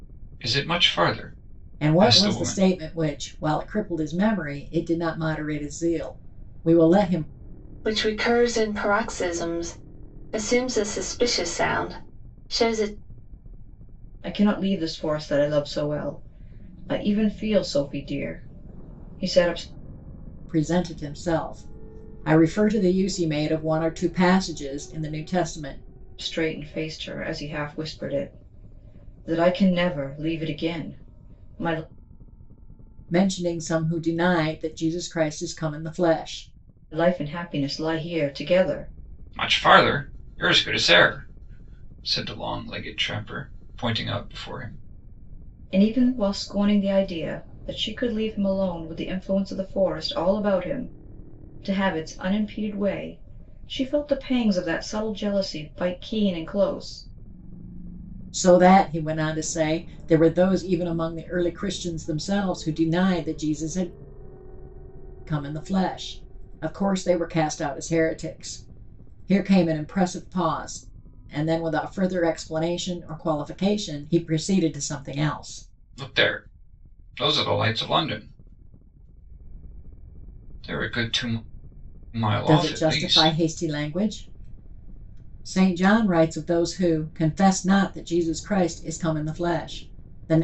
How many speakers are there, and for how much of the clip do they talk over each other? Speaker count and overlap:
4, about 2%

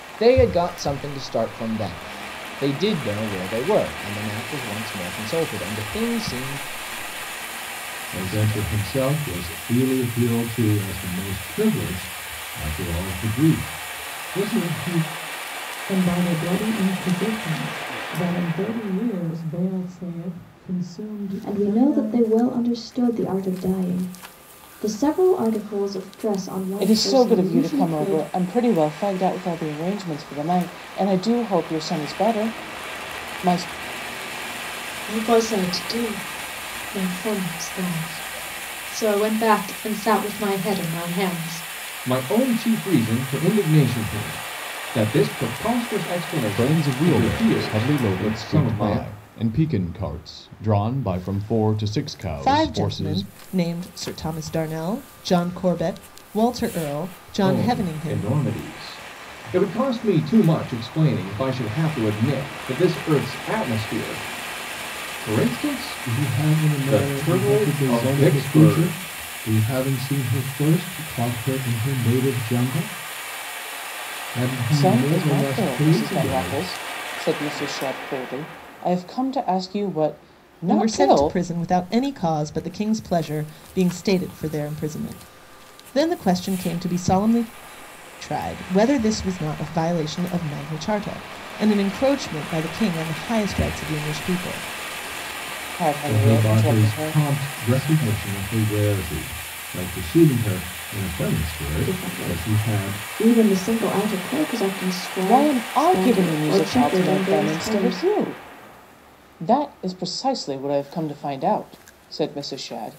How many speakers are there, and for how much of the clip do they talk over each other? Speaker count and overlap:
9, about 16%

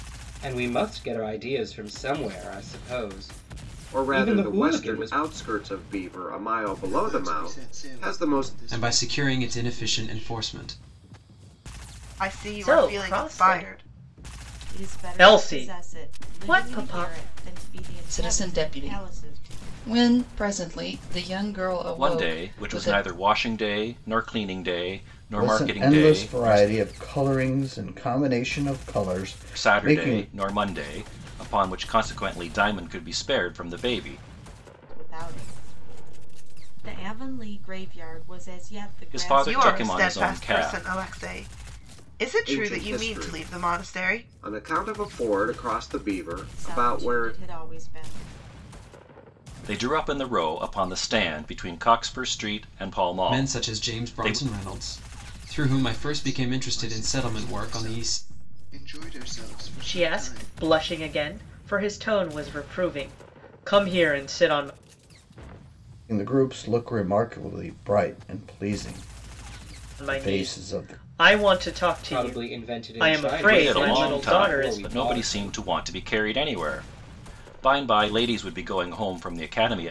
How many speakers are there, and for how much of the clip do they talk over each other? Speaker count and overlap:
10, about 33%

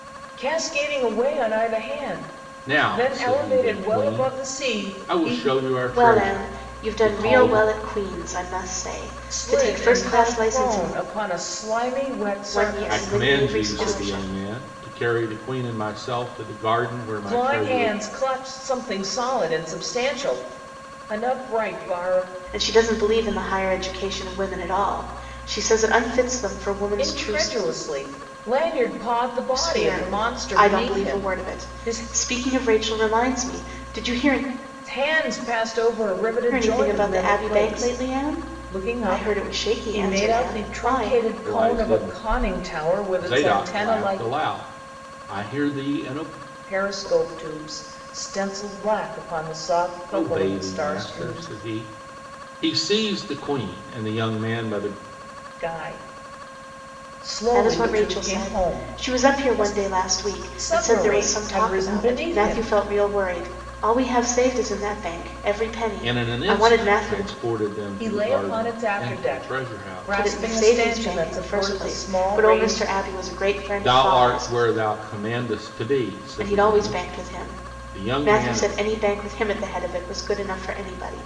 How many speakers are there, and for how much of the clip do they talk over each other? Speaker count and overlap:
3, about 42%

